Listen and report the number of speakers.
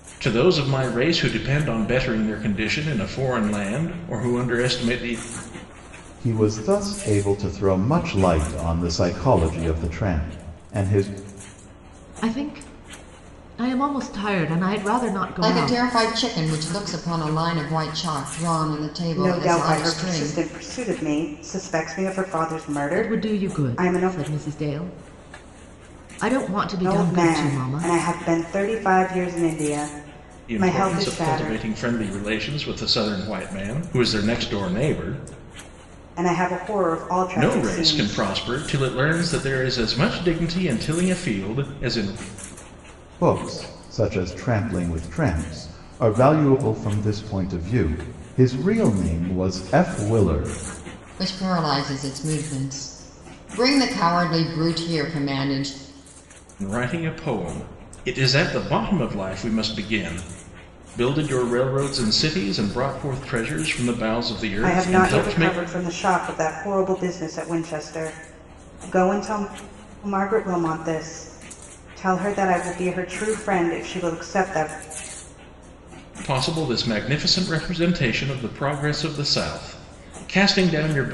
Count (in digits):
5